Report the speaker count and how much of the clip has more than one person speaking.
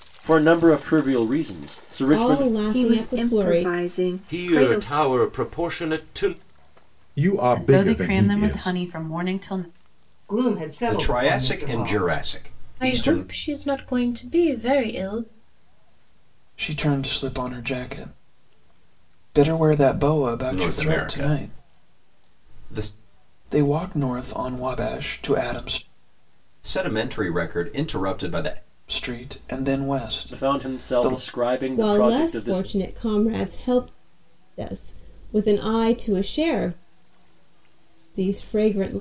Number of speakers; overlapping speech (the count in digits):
10, about 21%